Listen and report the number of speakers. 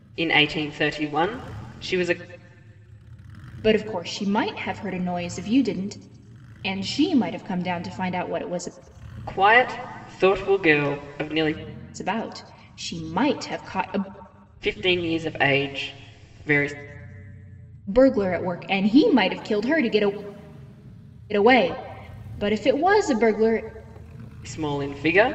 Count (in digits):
2